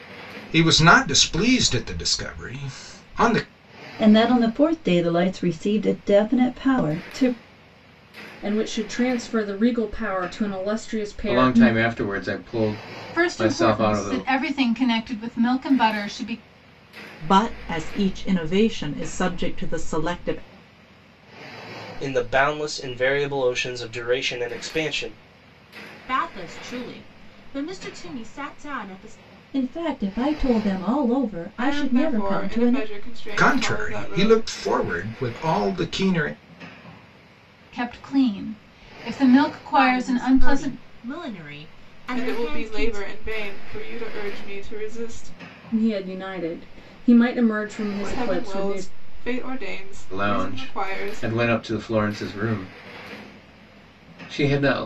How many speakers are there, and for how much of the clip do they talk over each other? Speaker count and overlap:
10, about 15%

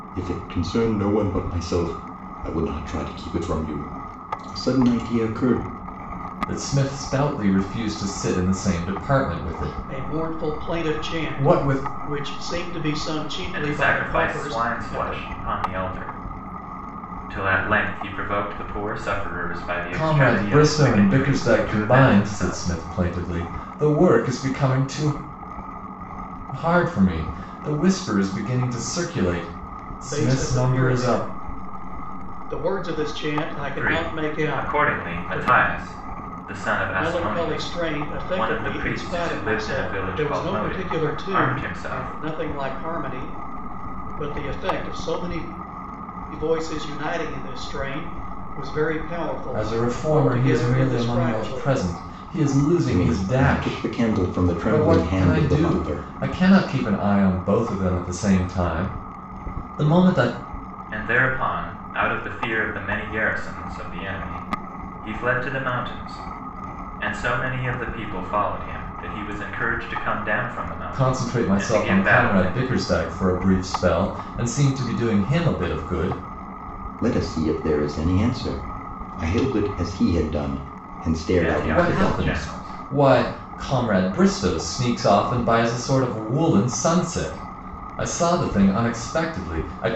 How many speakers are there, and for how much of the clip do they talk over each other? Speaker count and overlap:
4, about 27%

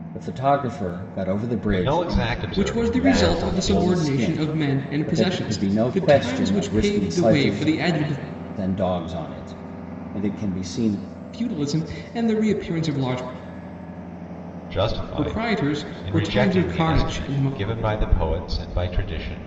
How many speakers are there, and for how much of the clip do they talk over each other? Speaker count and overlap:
3, about 42%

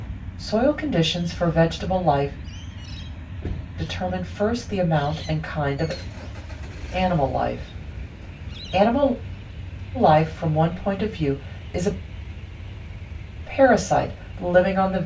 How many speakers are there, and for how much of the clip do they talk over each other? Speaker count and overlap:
1, no overlap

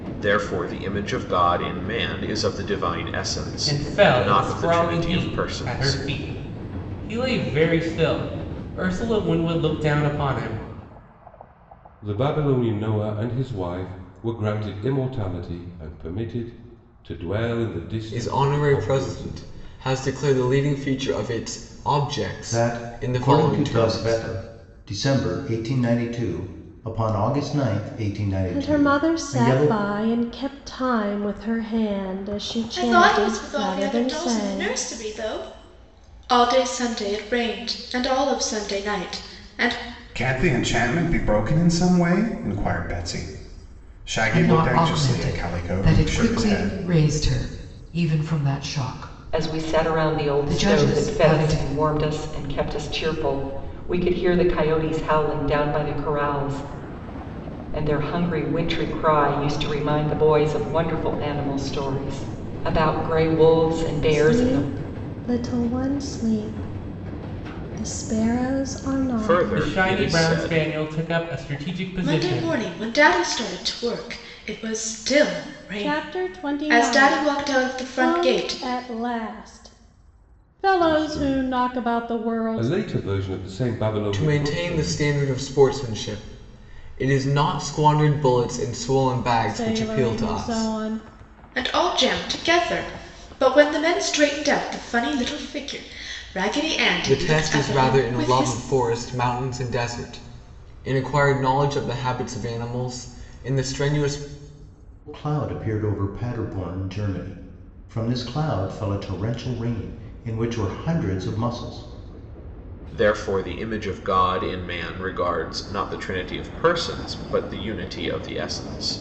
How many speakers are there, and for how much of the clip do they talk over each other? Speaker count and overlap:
10, about 21%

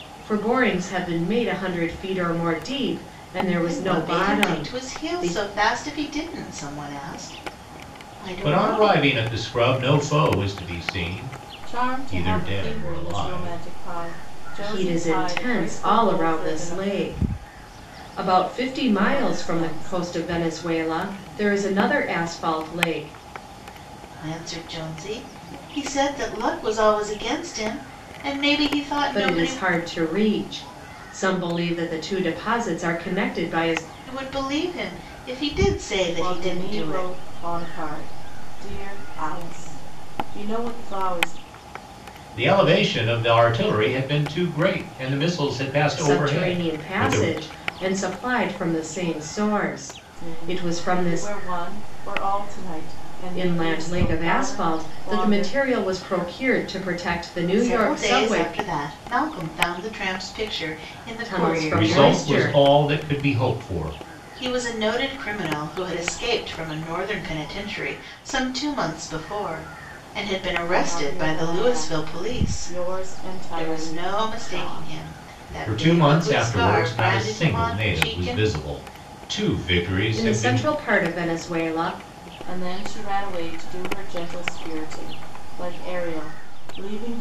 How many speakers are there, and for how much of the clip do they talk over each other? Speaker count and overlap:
4, about 27%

